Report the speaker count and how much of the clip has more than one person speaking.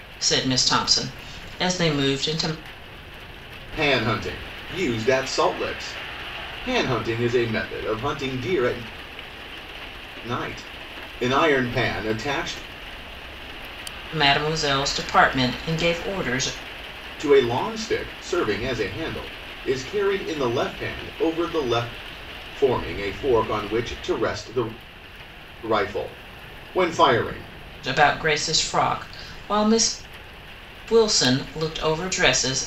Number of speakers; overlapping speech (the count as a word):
two, no overlap